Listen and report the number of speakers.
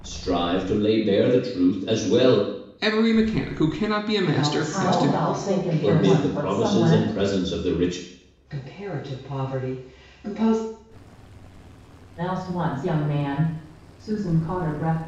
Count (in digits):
4